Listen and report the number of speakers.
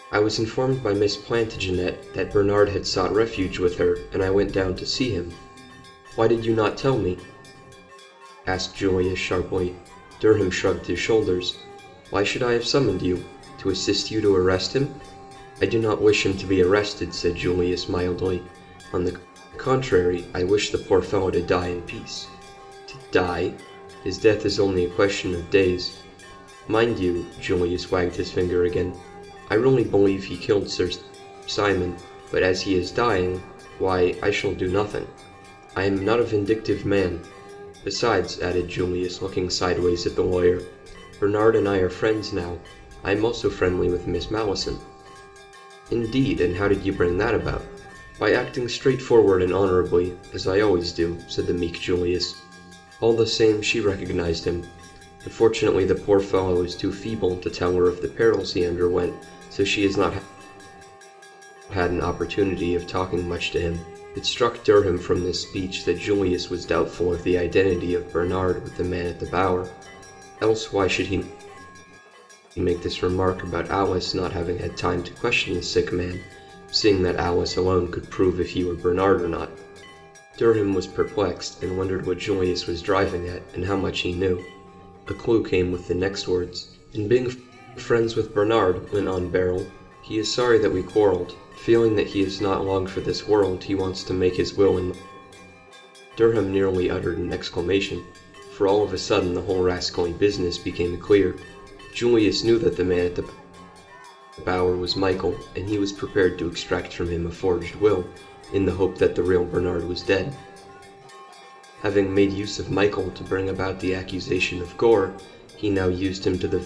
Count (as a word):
one